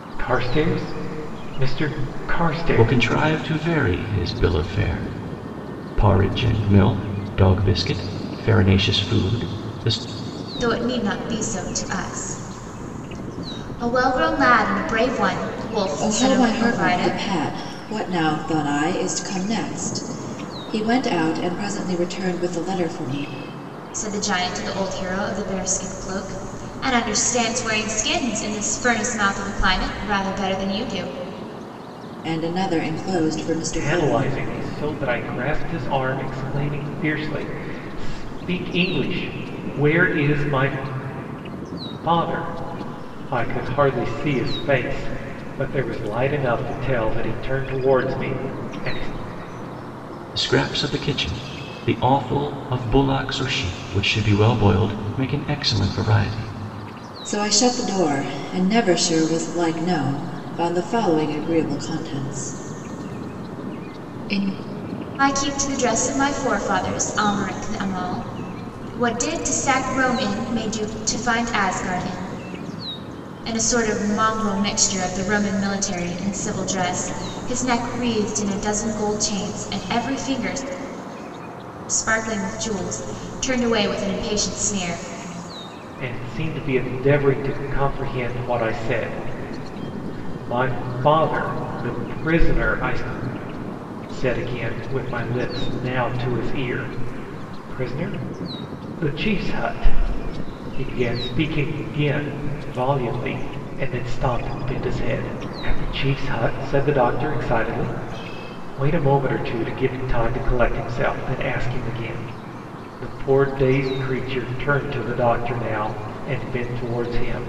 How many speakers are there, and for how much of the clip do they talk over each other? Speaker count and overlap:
4, about 2%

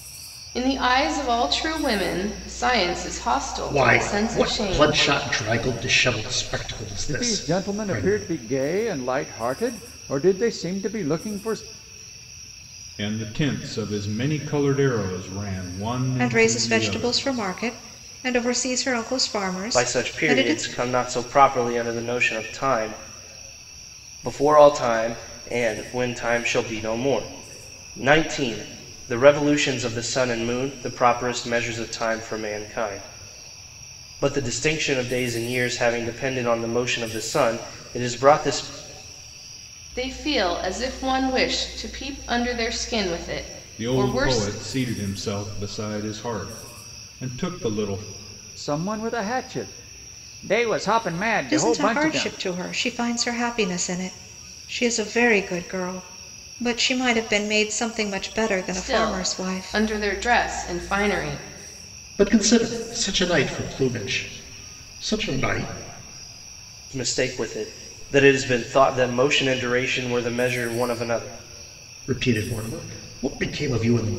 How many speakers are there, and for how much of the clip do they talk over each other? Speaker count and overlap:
6, about 10%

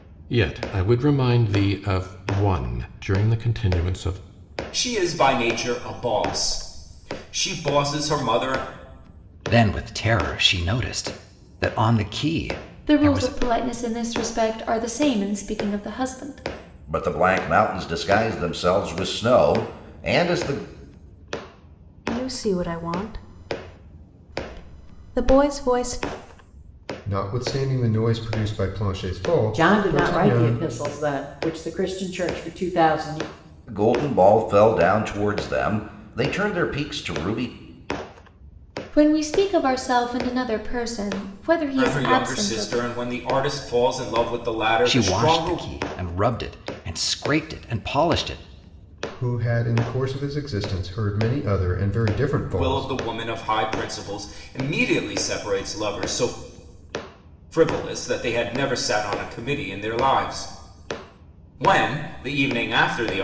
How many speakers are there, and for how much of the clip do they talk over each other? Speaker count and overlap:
8, about 6%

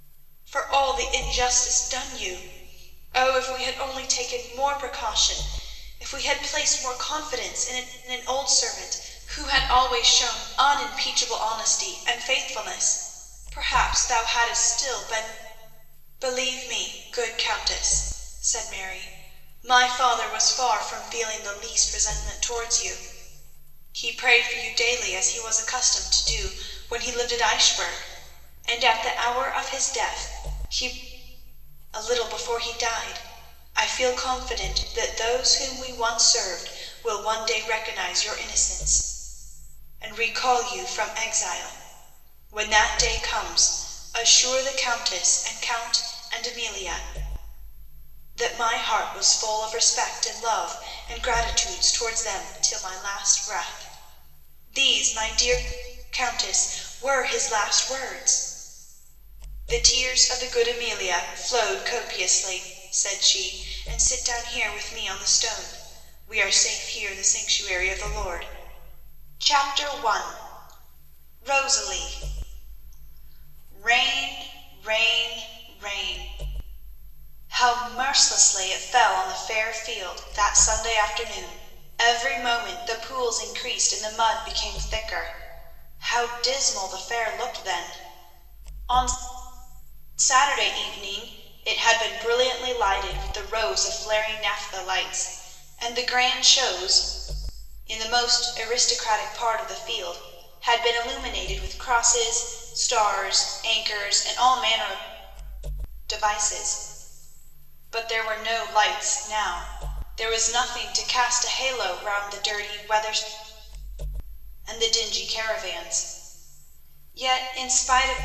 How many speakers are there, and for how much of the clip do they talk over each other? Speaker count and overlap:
1, no overlap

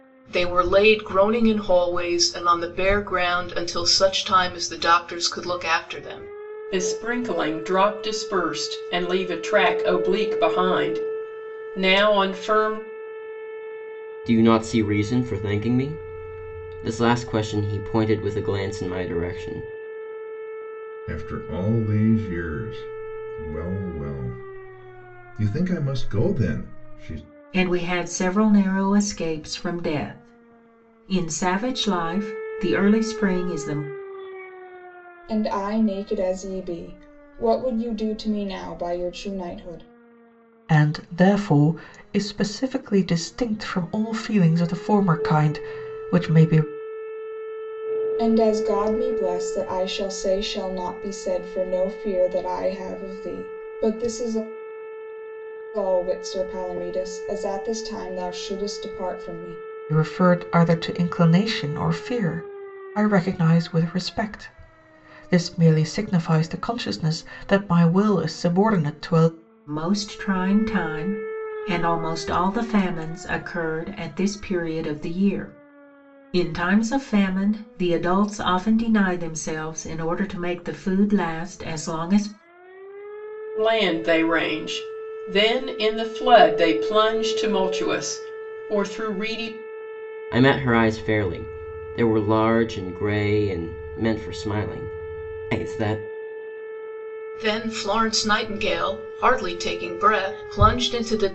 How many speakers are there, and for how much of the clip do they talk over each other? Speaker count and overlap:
7, no overlap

